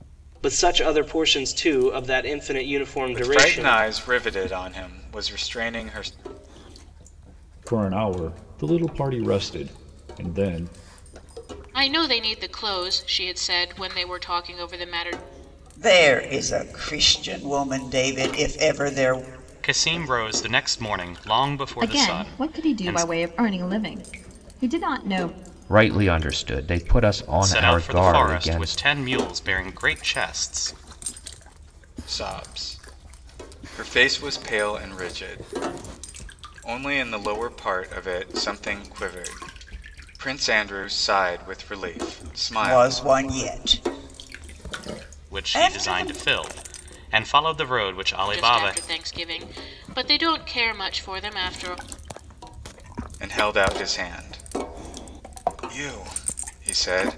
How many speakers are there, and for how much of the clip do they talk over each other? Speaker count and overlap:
8, about 9%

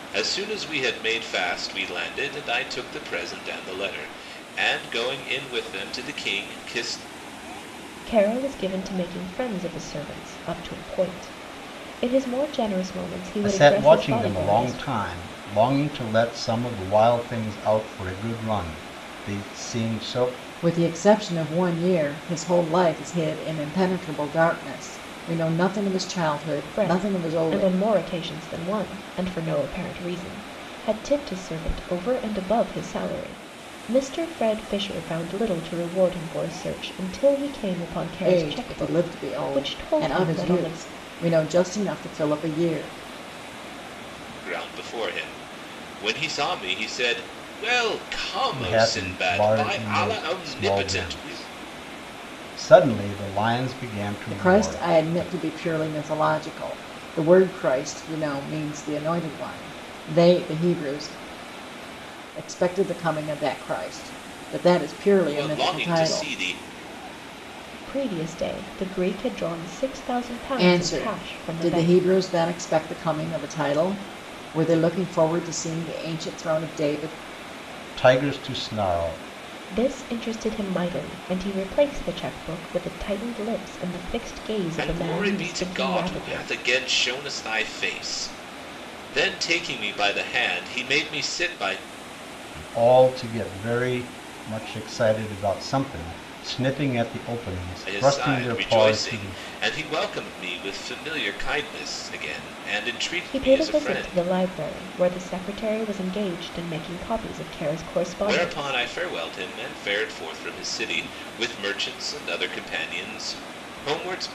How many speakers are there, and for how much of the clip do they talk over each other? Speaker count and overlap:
4, about 14%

